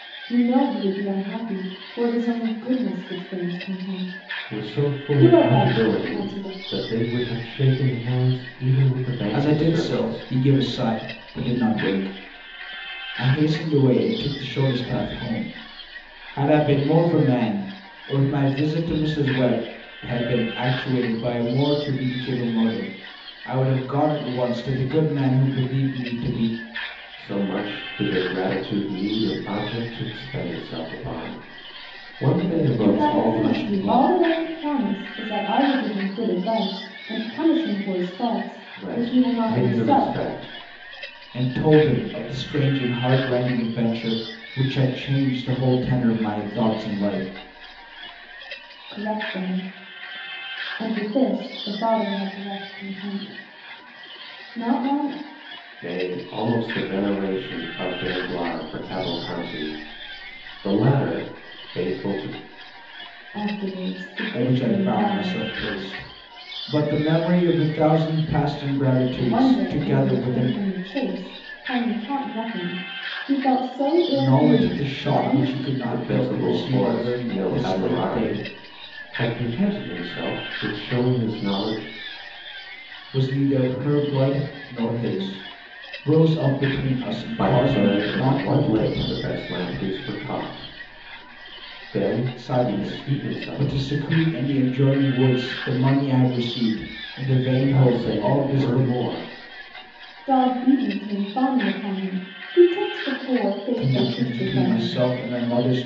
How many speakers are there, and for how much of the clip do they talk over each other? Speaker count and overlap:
3, about 18%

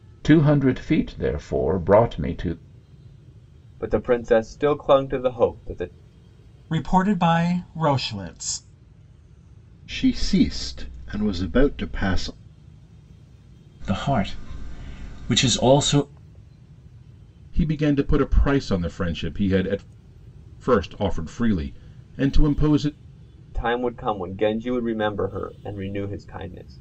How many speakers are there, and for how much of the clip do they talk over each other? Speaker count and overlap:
6, no overlap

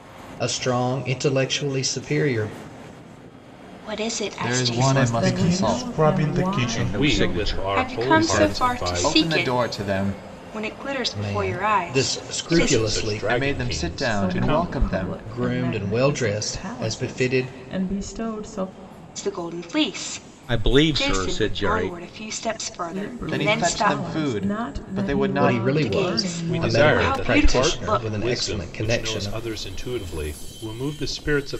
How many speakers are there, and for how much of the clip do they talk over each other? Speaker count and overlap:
7, about 62%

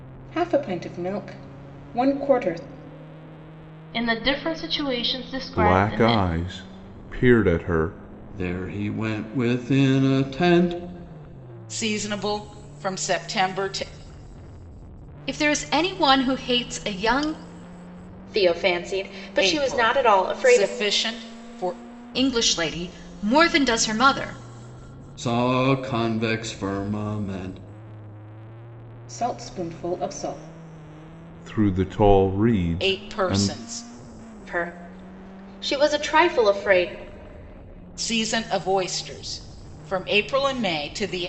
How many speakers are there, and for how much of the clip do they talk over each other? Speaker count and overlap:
7, about 7%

